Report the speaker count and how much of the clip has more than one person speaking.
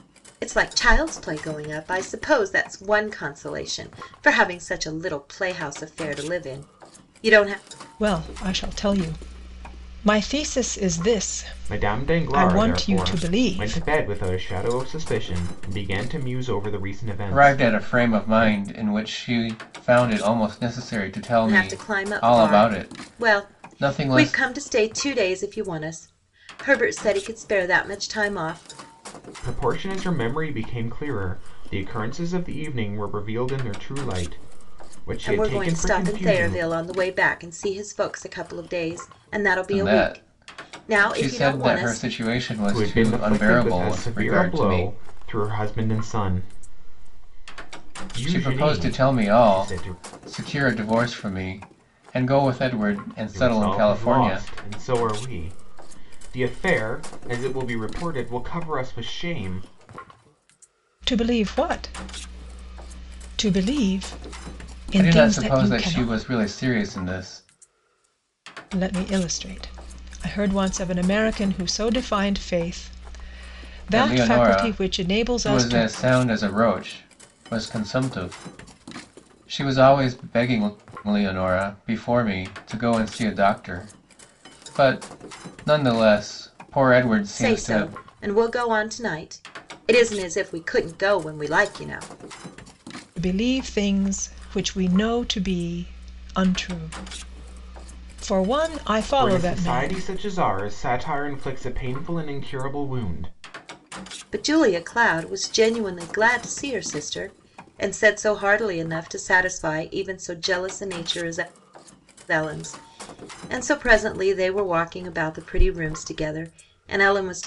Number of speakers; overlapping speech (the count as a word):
four, about 17%